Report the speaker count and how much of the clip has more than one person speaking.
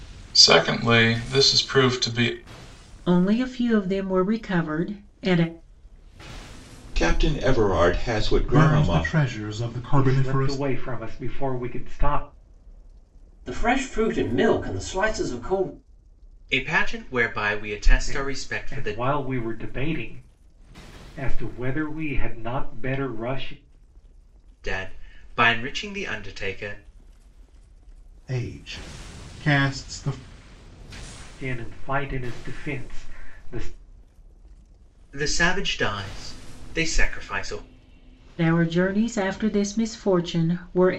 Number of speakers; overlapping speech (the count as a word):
seven, about 6%